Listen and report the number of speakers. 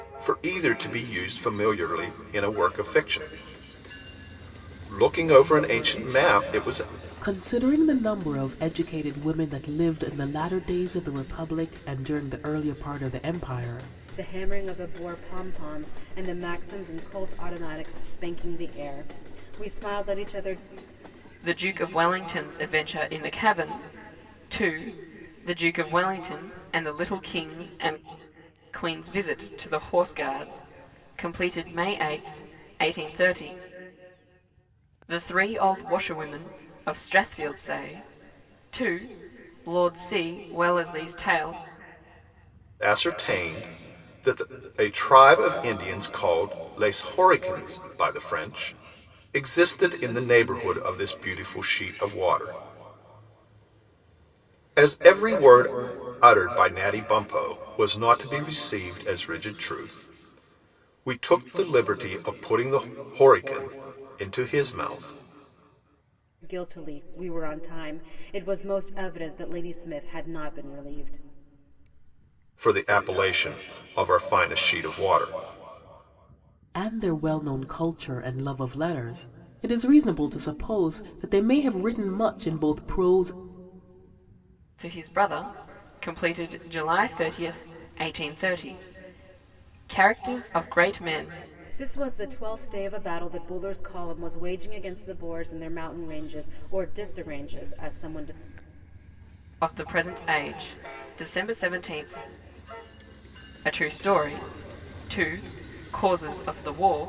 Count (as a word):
four